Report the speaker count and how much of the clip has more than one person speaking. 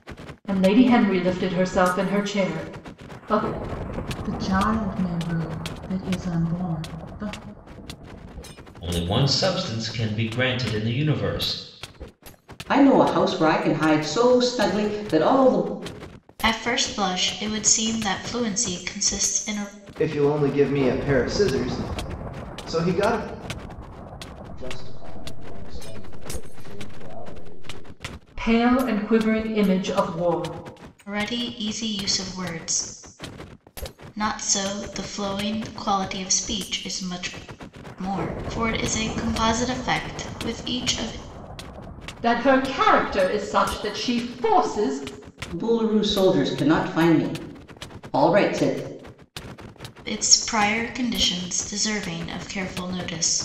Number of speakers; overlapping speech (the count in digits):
7, no overlap